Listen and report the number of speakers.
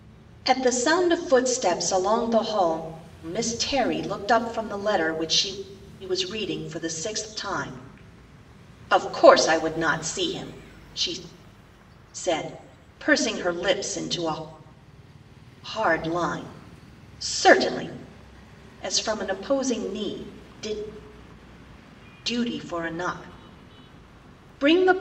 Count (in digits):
1